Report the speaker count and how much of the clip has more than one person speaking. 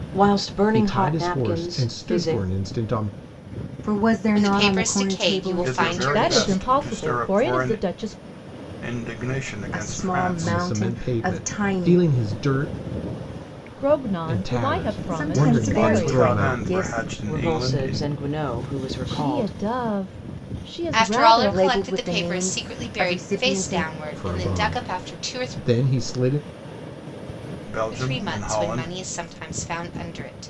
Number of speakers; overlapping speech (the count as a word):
six, about 57%